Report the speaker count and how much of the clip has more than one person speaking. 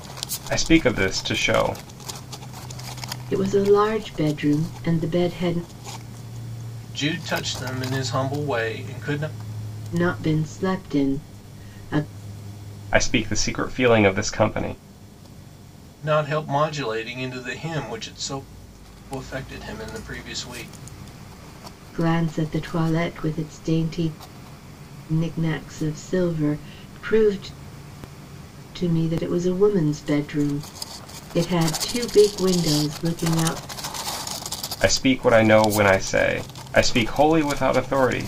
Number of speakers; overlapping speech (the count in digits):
3, no overlap